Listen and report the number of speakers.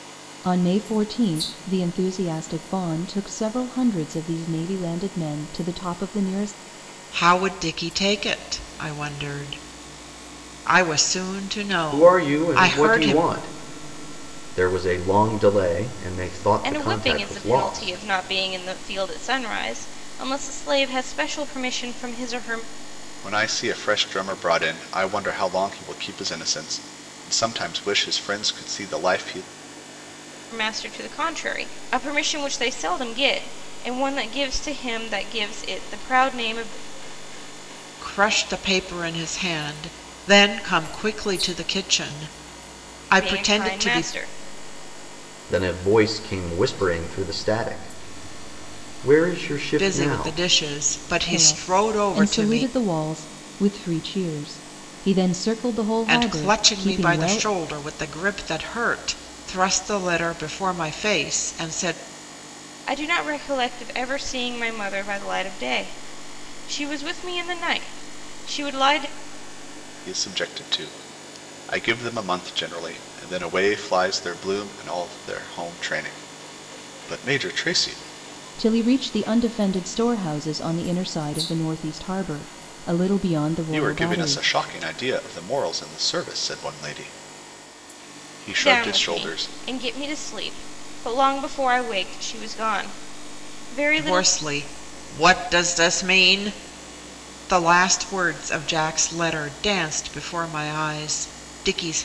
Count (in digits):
5